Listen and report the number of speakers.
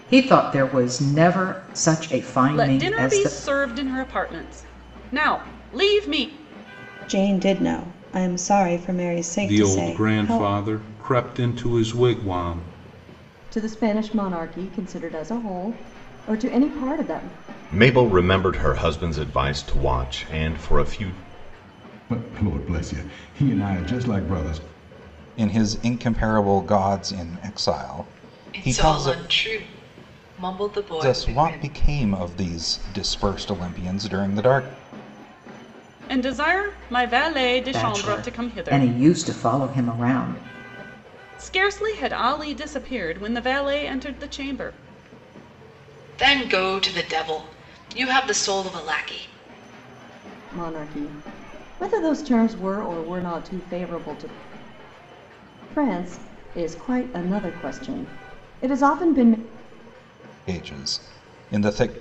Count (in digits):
9